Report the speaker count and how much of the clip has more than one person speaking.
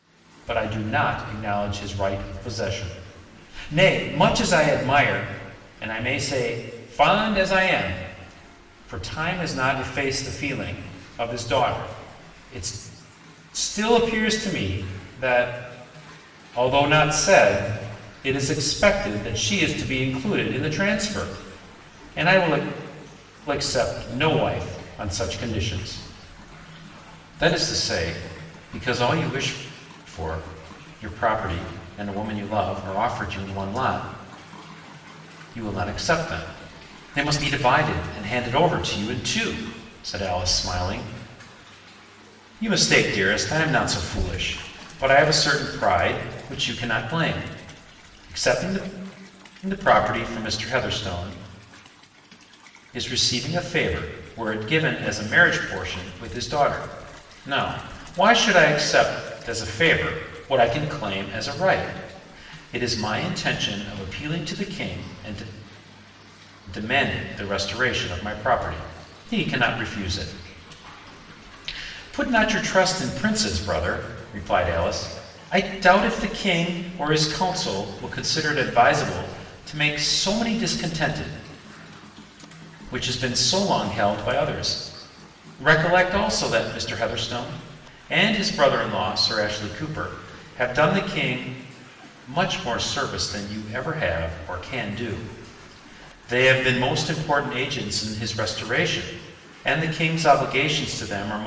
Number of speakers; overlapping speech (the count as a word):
one, no overlap